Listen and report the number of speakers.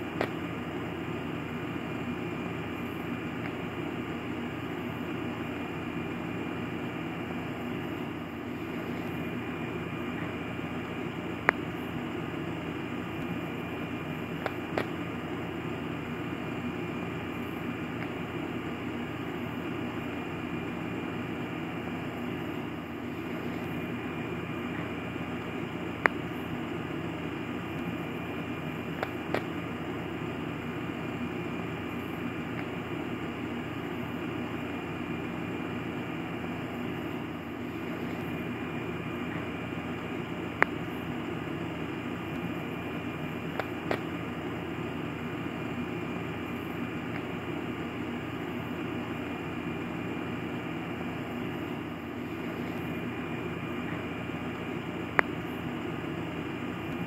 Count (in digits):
0